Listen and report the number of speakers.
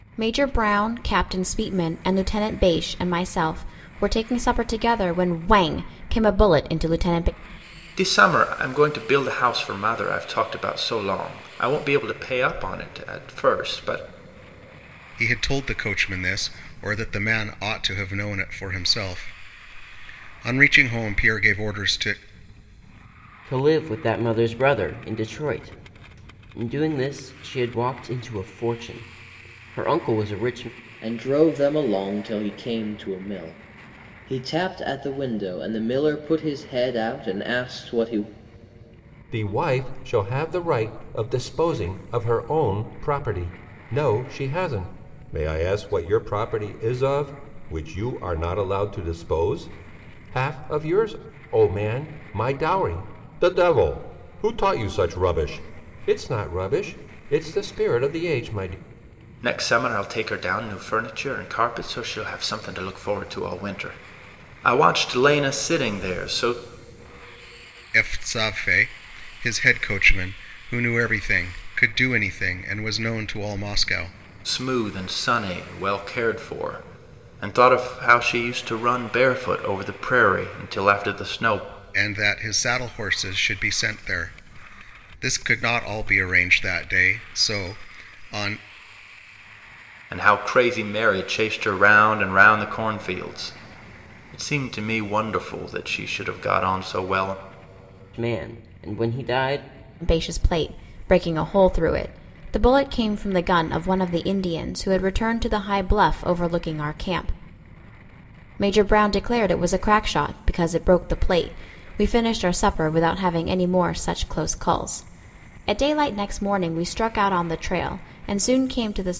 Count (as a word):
six